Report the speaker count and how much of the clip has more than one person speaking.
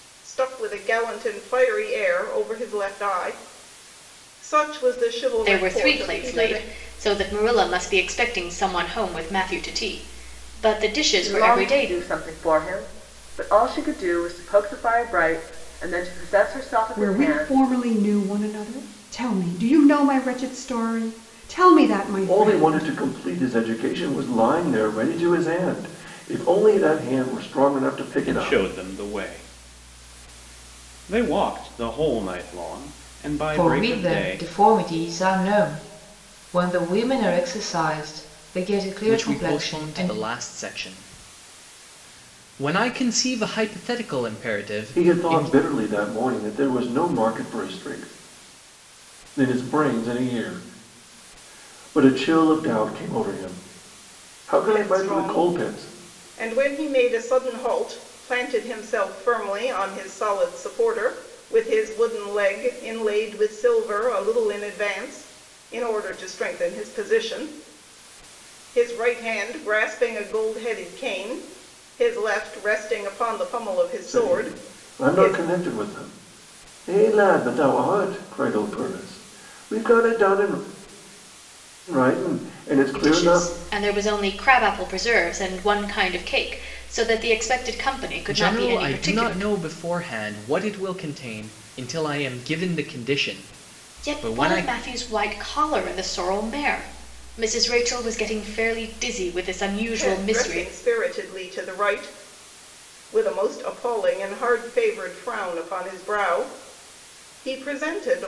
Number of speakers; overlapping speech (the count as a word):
eight, about 12%